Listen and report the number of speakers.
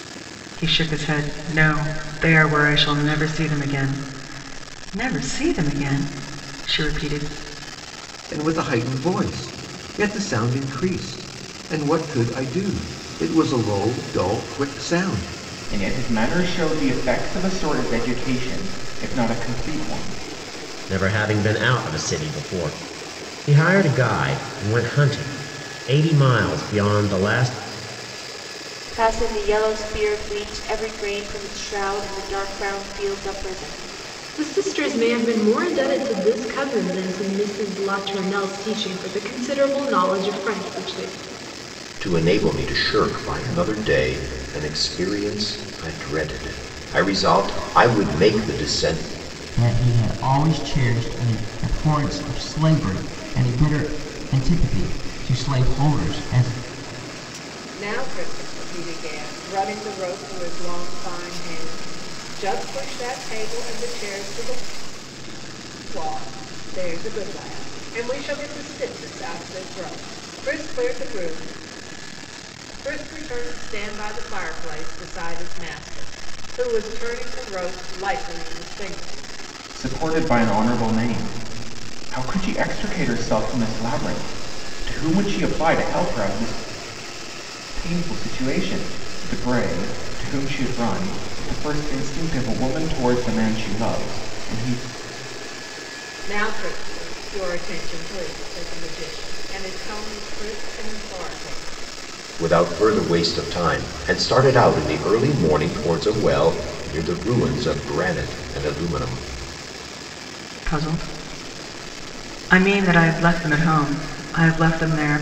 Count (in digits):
9